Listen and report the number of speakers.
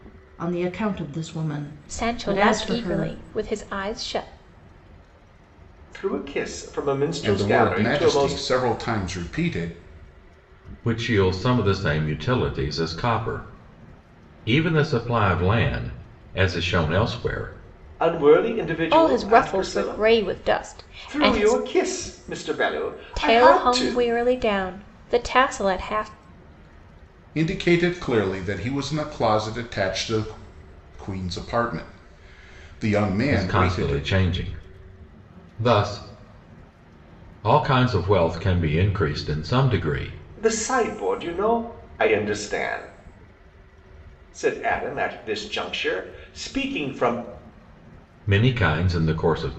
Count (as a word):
five